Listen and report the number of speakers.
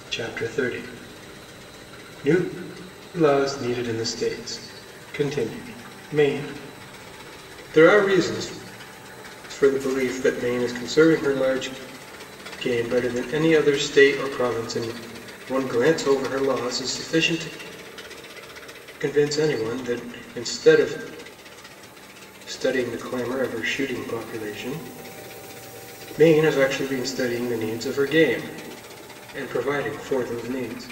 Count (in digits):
1